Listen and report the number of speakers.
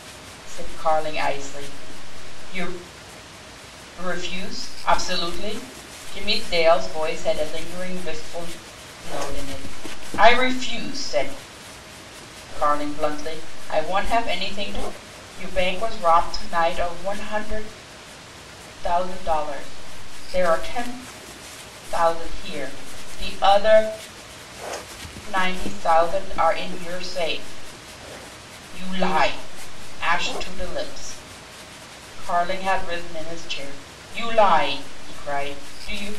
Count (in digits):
1